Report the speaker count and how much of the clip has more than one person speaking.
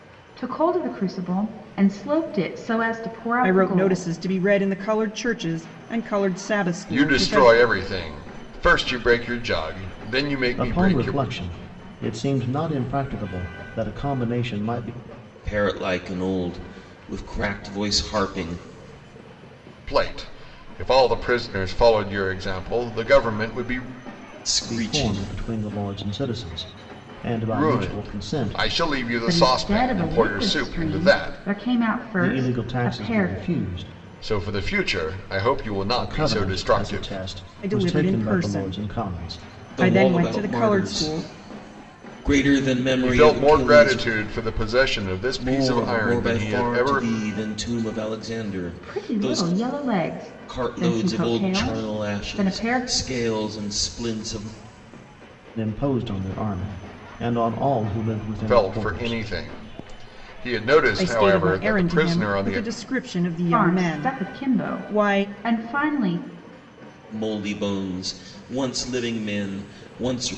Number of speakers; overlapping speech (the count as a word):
five, about 32%